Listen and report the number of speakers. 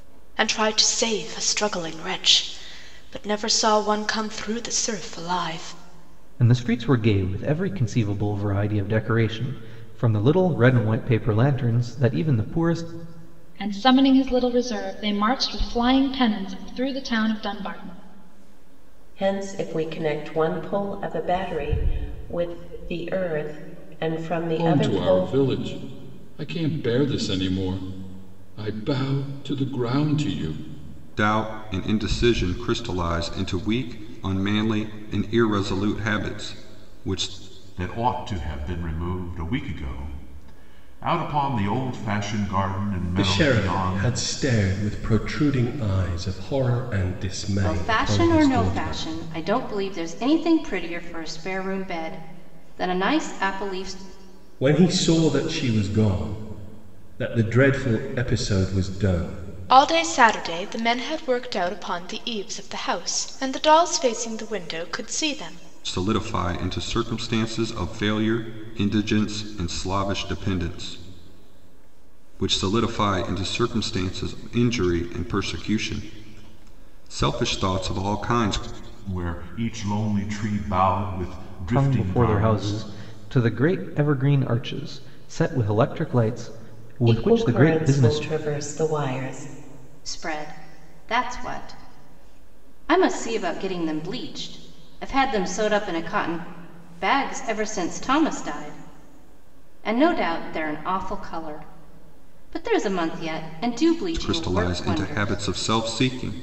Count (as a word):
nine